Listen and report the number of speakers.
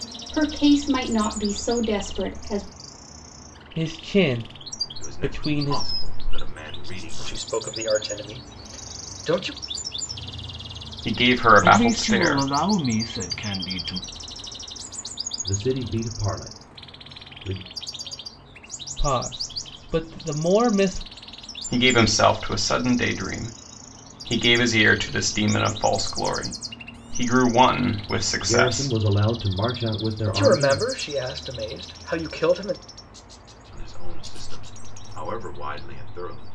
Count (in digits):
7